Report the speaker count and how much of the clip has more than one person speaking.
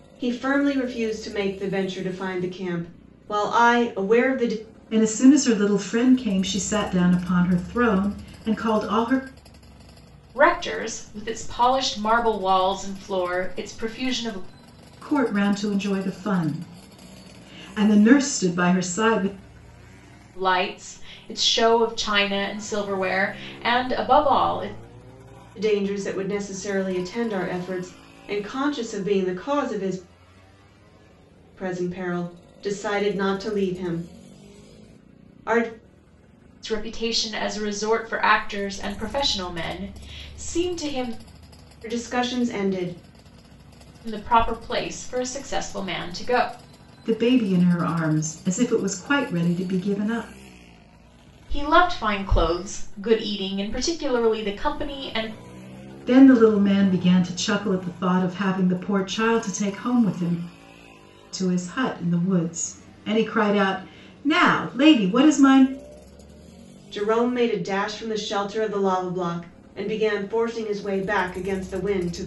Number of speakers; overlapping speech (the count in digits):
3, no overlap